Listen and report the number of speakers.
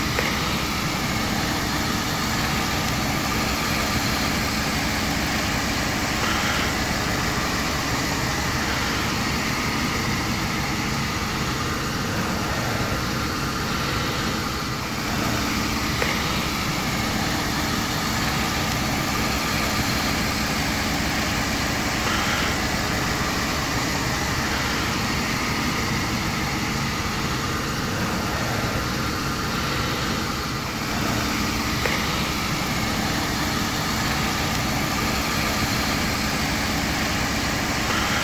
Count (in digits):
0